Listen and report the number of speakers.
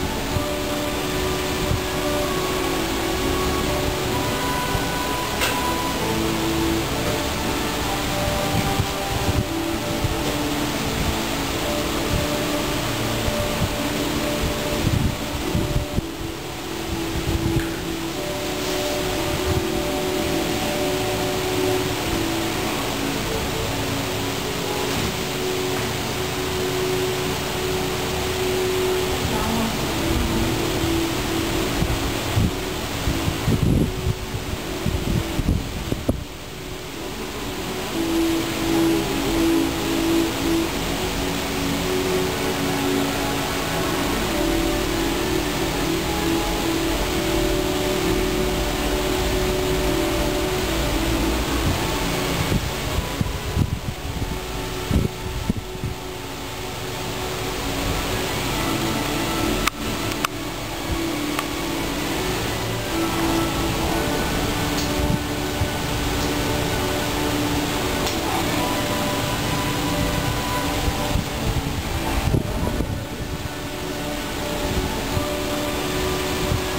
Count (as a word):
zero